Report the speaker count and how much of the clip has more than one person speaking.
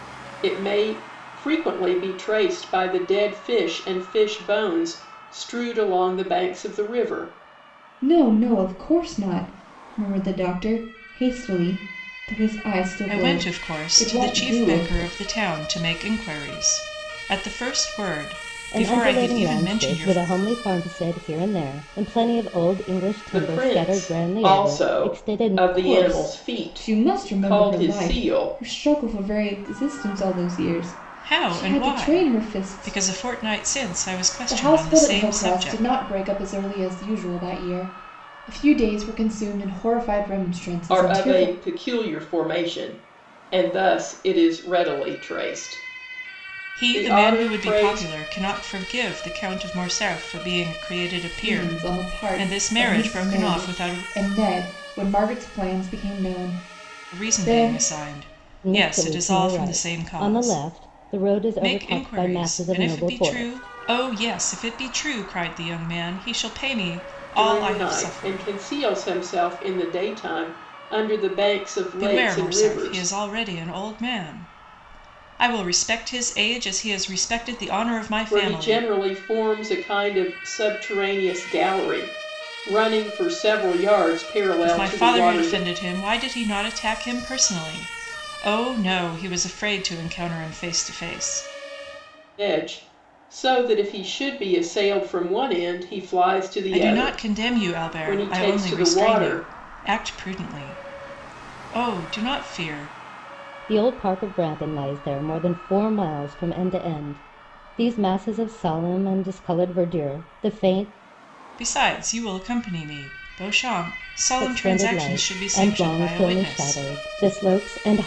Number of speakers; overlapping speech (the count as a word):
four, about 26%